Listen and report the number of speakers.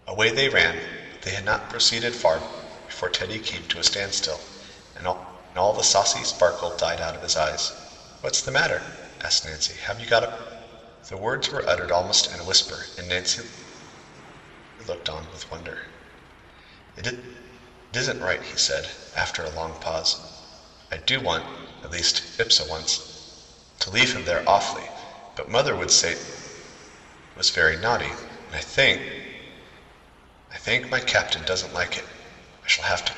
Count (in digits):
1